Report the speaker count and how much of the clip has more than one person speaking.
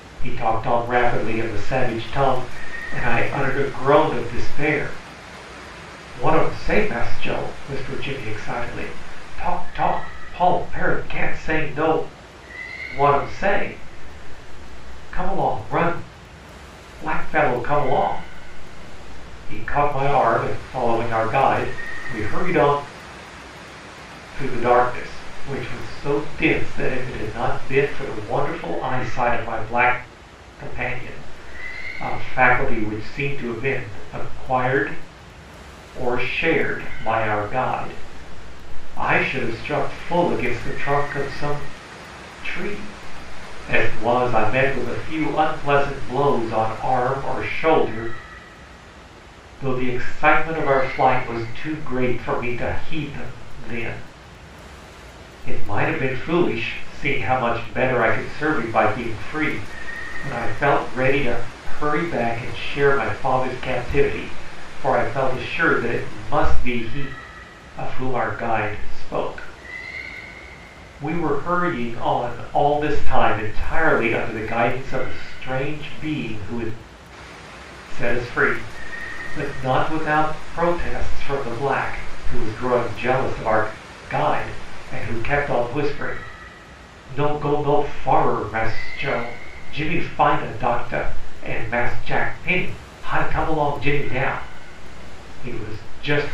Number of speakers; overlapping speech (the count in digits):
1, no overlap